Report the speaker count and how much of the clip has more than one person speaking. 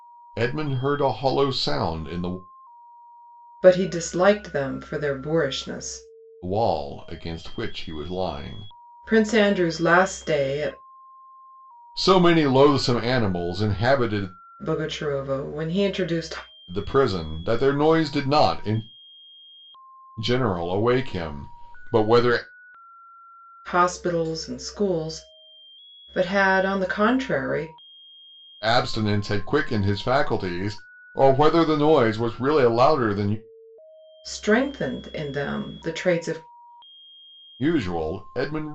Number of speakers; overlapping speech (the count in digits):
2, no overlap